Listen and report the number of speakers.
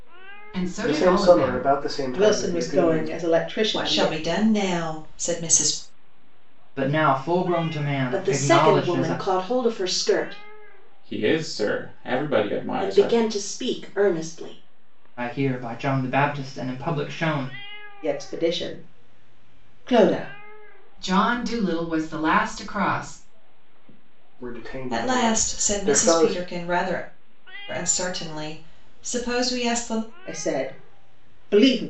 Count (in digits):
7